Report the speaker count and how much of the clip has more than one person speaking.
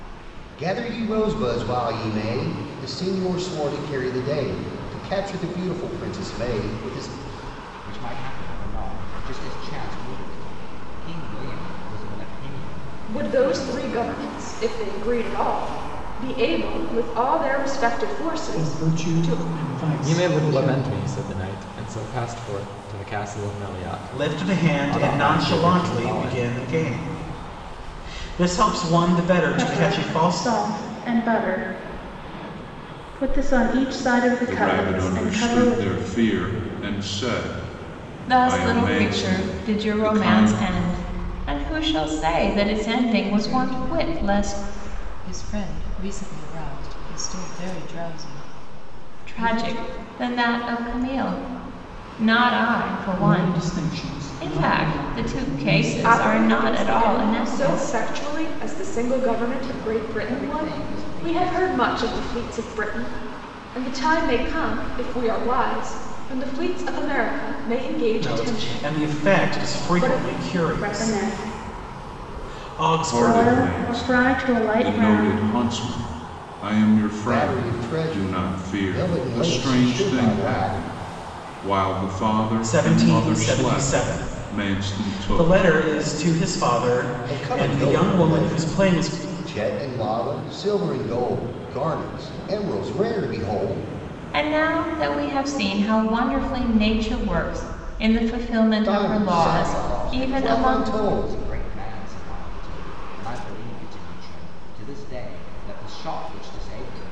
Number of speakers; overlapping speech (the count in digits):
10, about 35%